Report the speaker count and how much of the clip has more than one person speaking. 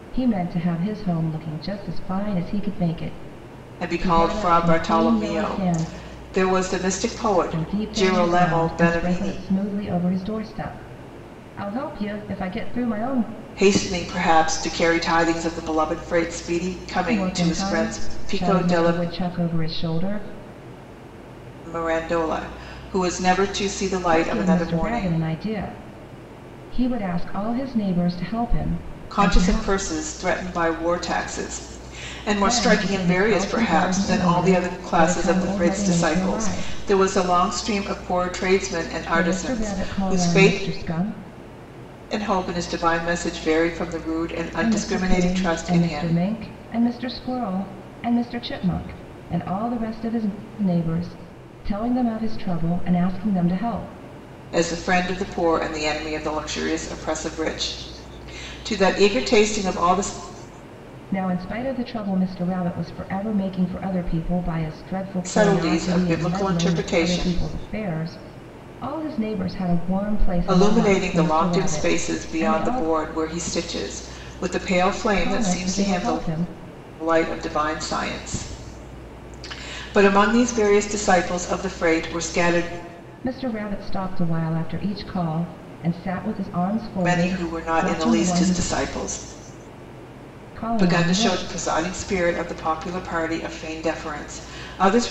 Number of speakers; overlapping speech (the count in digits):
2, about 25%